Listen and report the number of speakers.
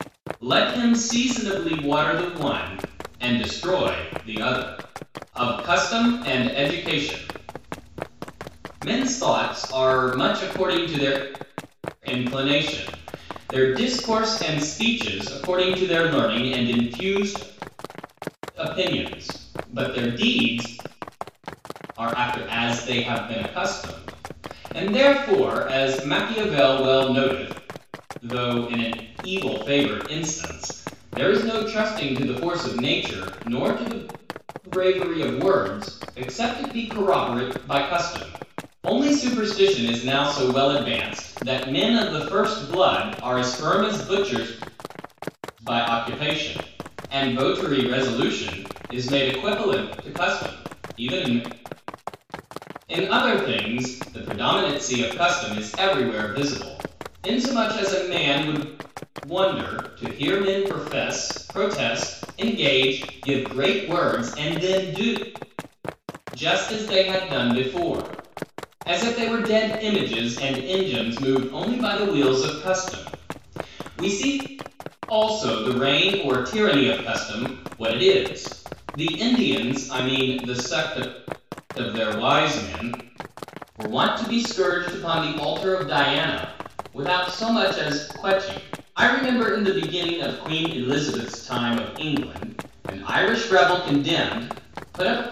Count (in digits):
1